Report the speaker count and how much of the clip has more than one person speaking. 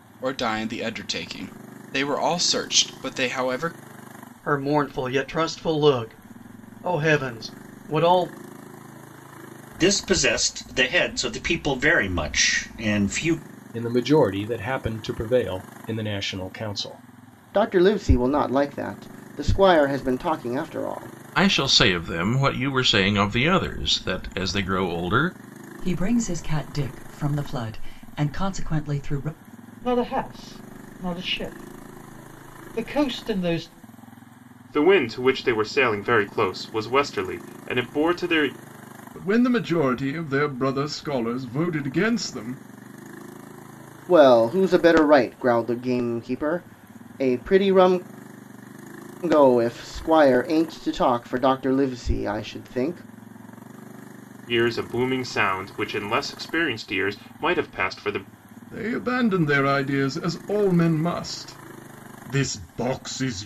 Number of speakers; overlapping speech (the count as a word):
ten, no overlap